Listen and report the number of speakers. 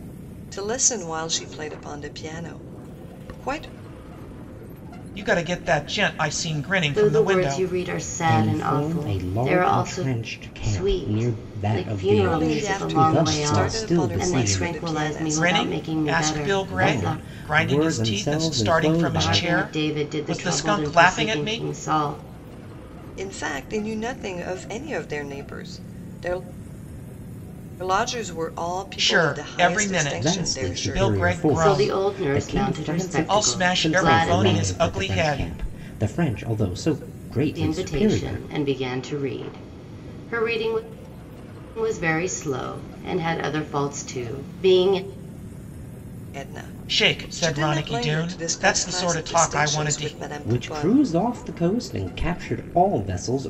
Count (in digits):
4